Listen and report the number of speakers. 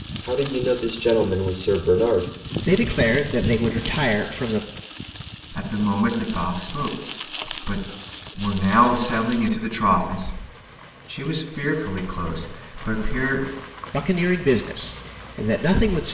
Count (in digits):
3